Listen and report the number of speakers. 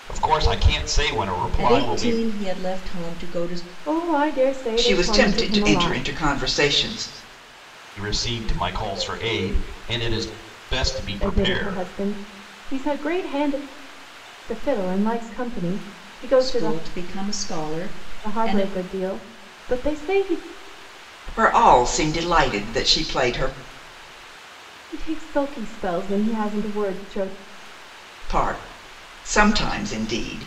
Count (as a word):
four